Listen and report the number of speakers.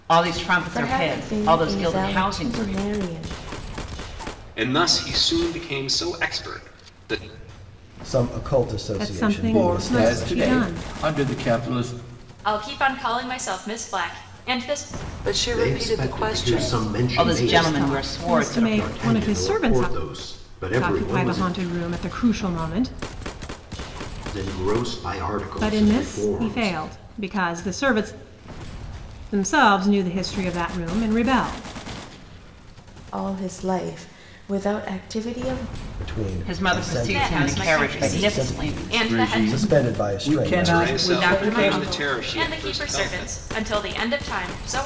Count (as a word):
nine